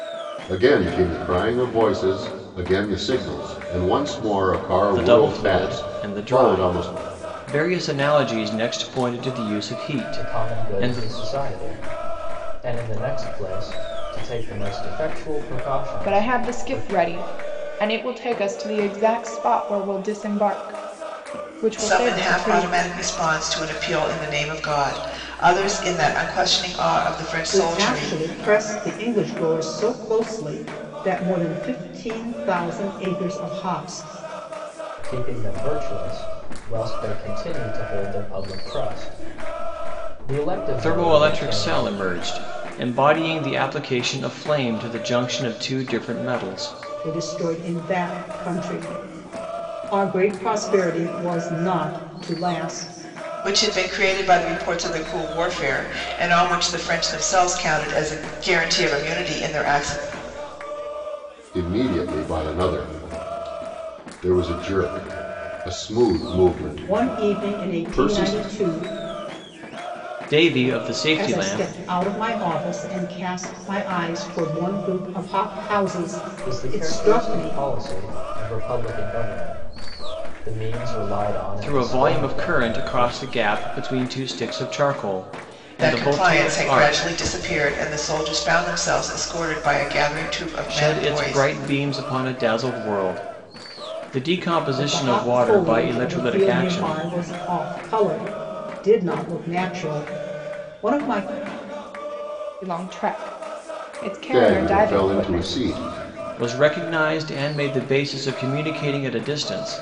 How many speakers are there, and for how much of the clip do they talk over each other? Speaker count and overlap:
6, about 16%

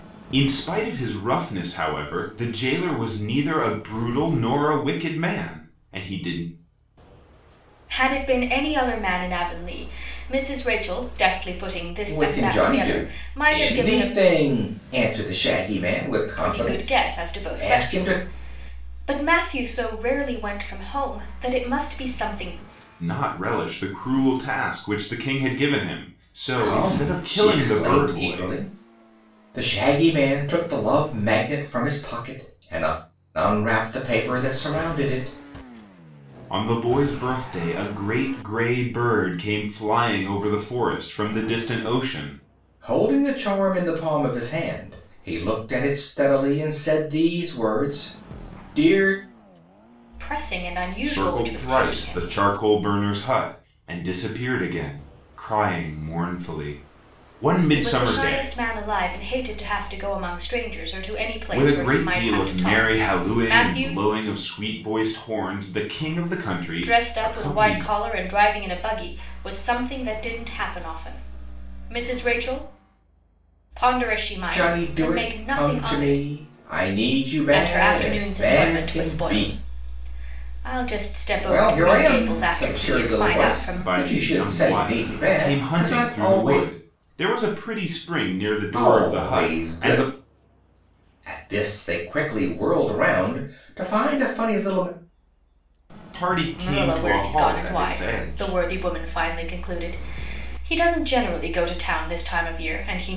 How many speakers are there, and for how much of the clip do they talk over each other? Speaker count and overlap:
3, about 23%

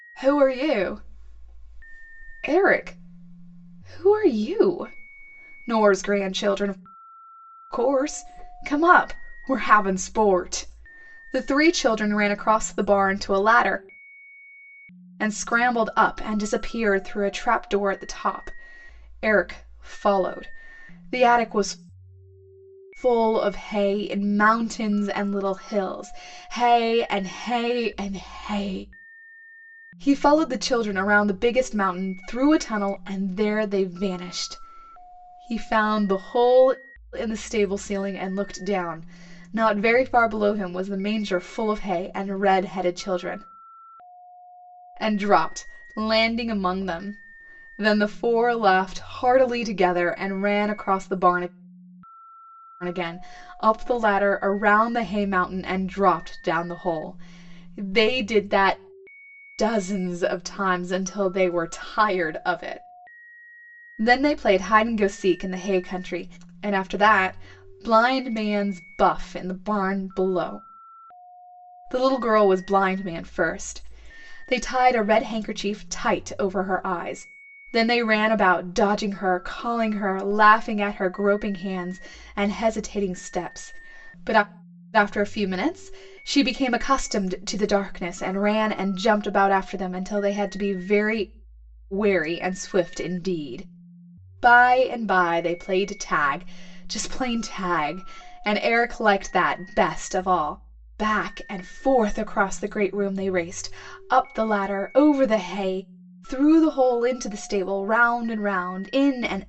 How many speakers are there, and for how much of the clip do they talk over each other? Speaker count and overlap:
1, no overlap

